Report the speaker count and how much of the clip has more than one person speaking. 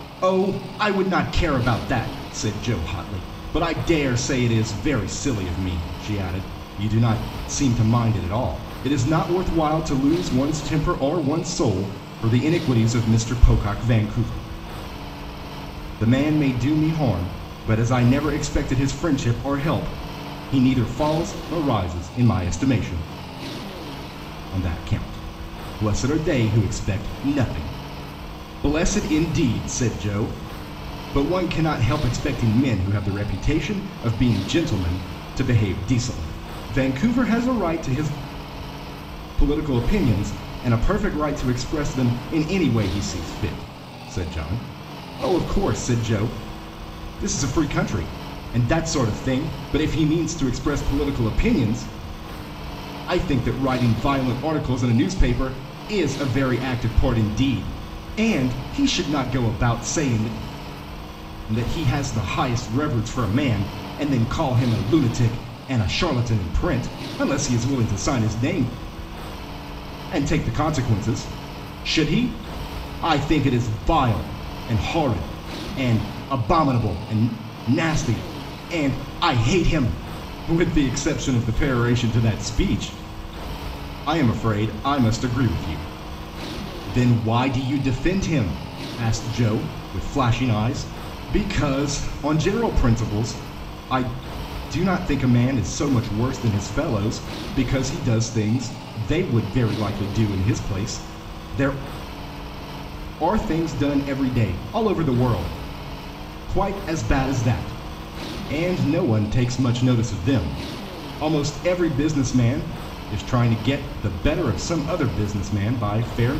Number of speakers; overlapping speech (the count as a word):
one, no overlap